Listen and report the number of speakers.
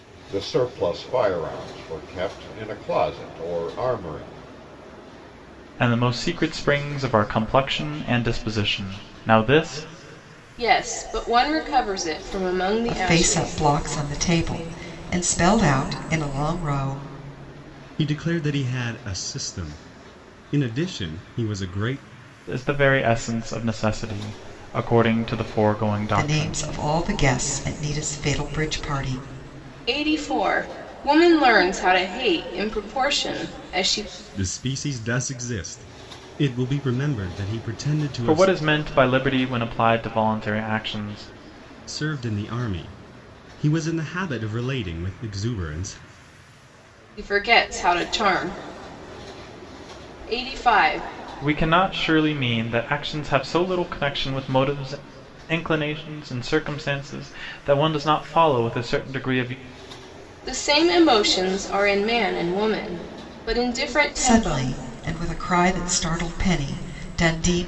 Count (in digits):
5